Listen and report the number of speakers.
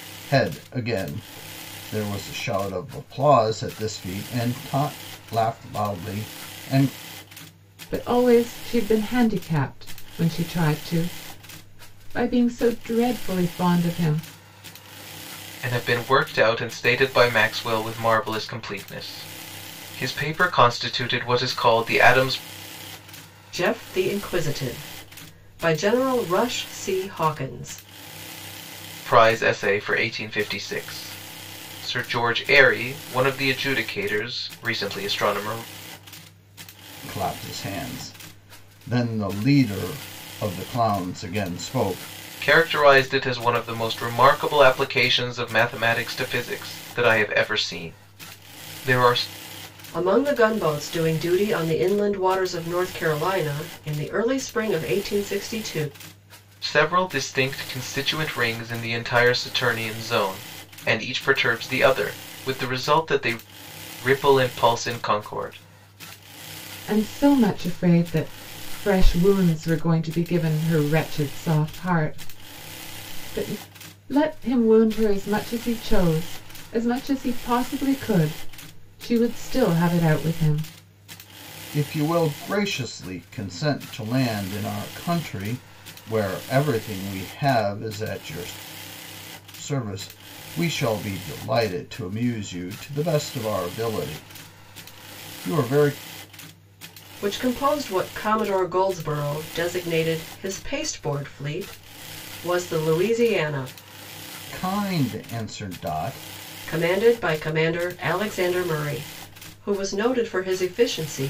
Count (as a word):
four